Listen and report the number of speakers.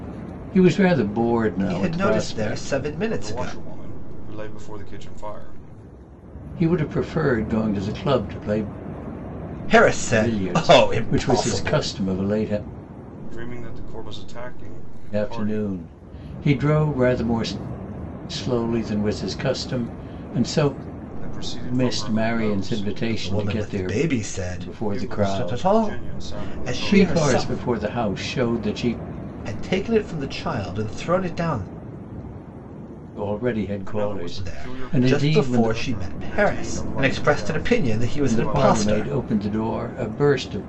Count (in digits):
3